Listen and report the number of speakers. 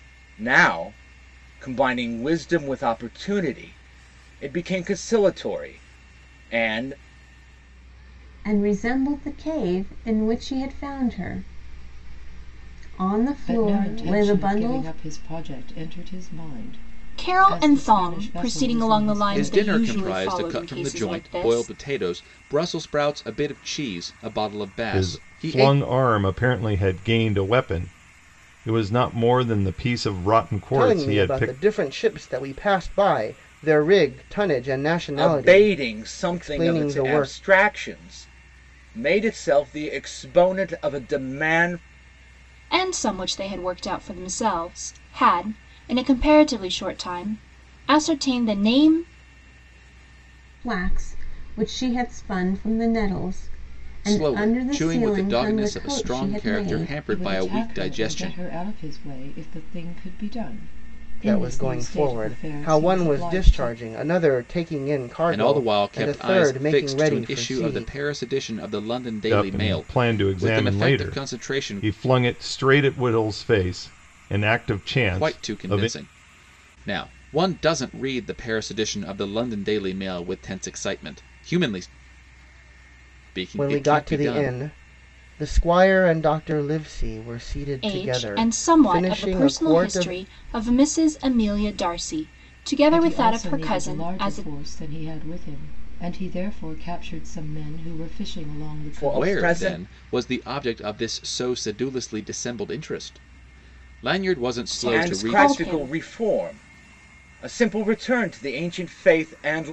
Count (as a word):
seven